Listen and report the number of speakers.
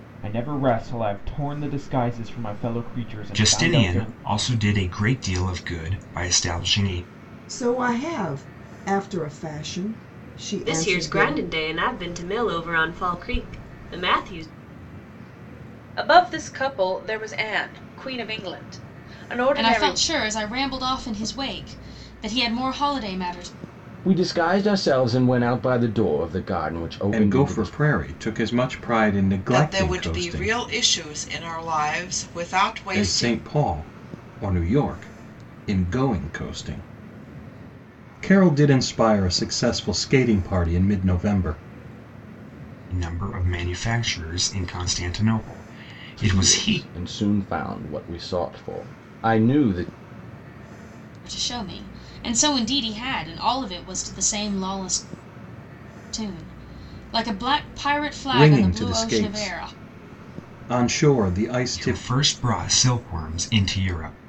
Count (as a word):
nine